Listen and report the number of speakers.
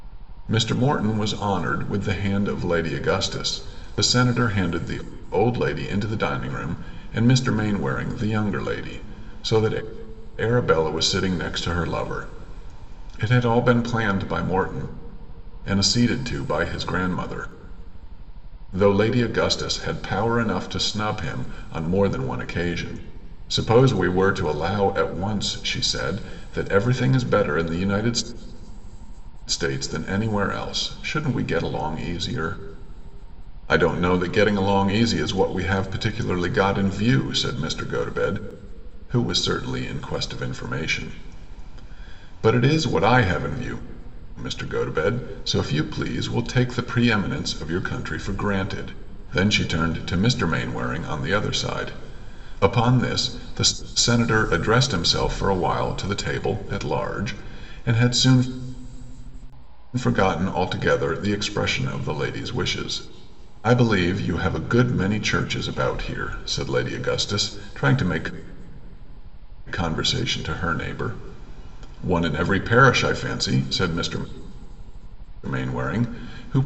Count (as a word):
one